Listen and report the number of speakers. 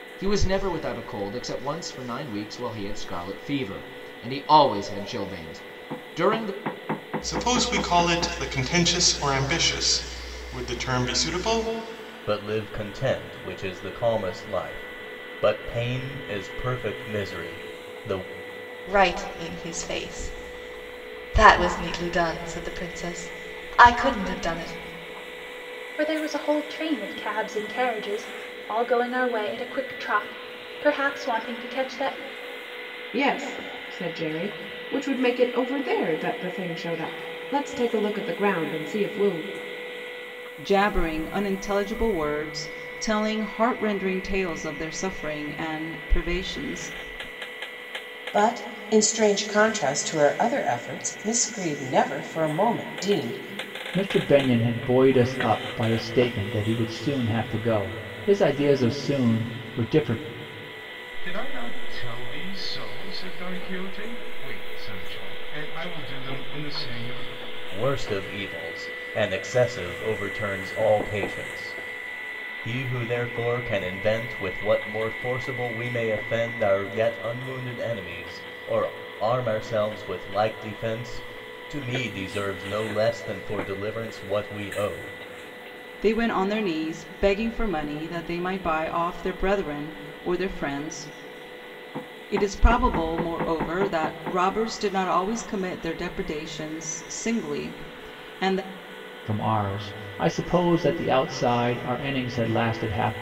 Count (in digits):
10